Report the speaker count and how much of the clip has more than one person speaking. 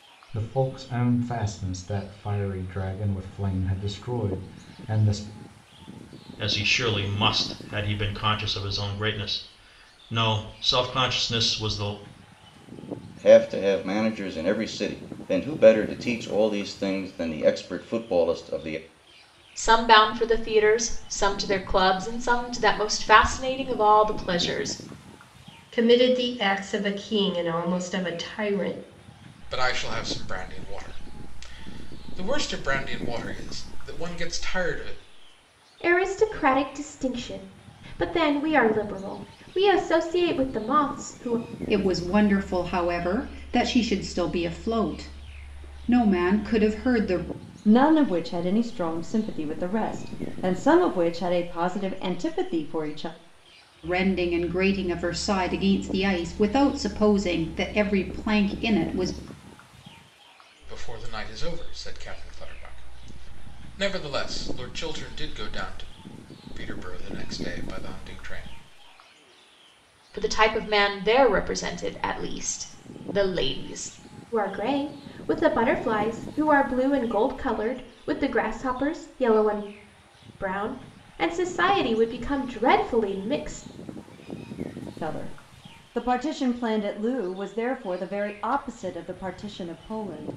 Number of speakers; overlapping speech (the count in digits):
9, no overlap